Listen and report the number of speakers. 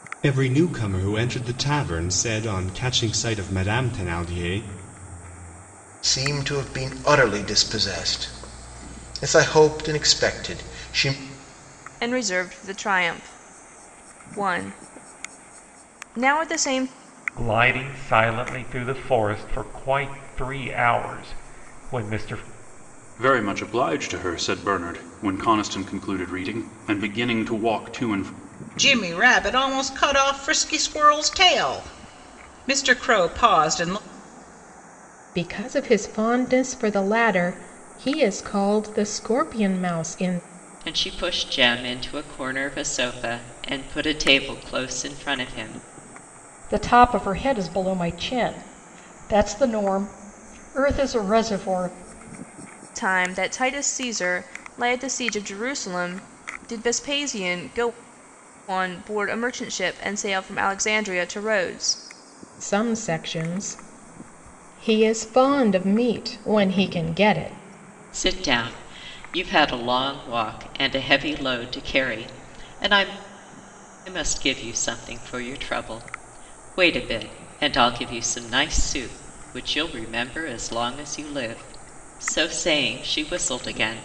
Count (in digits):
9